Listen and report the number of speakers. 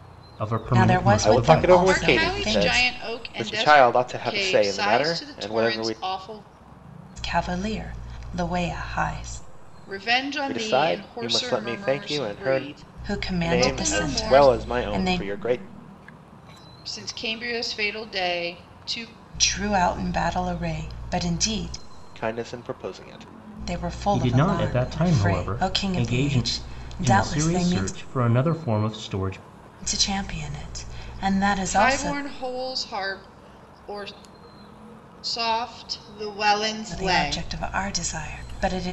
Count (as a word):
four